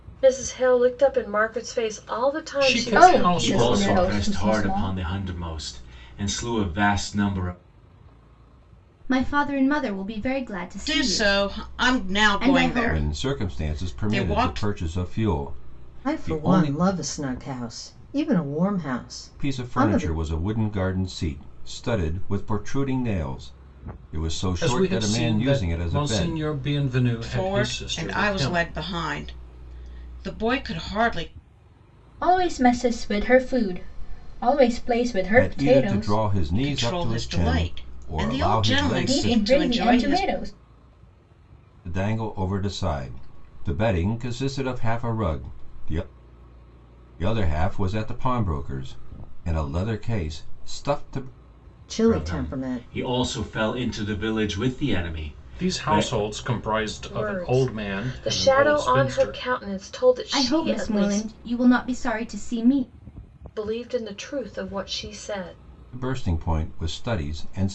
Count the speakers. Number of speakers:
8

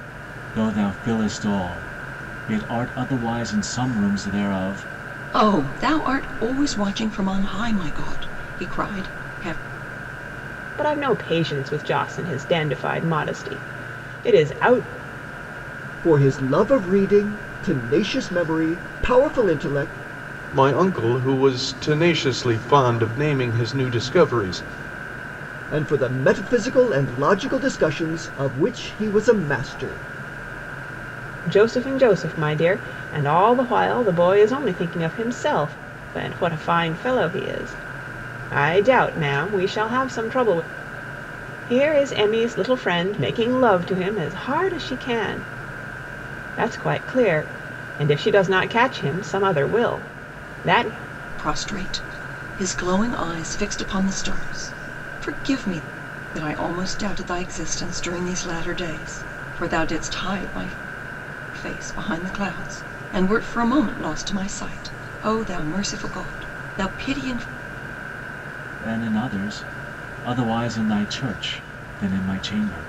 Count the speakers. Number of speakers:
5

